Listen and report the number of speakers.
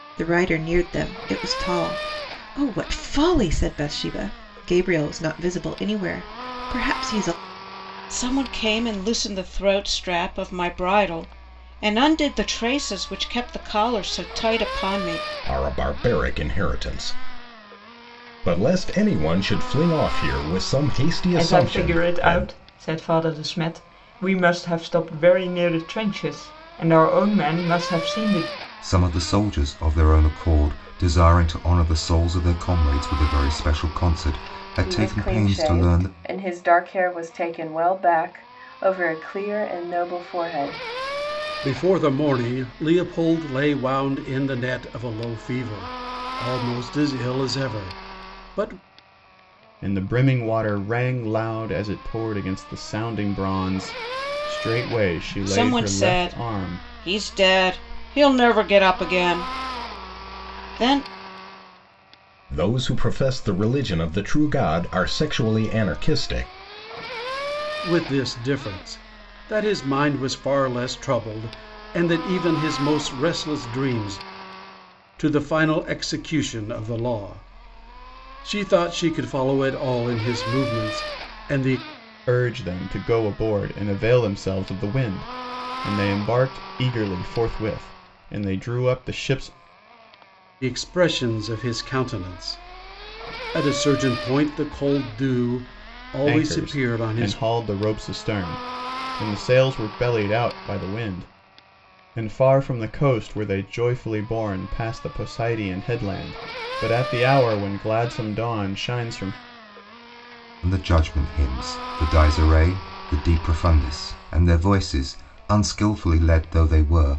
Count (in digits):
8